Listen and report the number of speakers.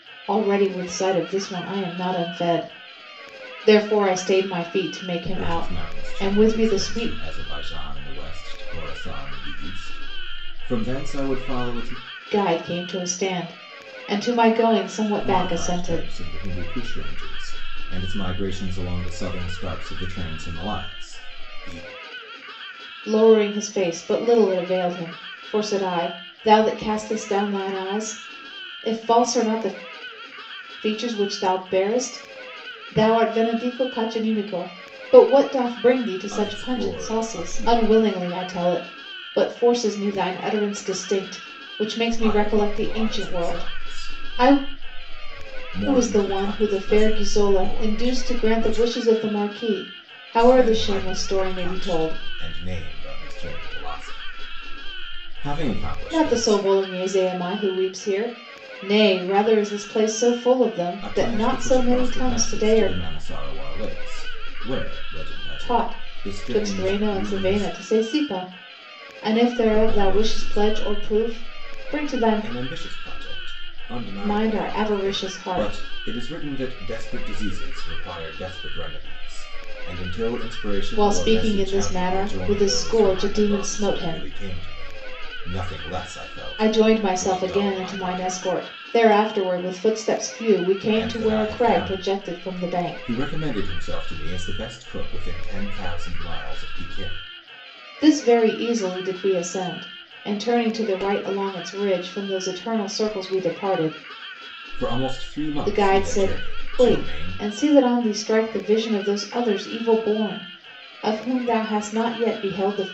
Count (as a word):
two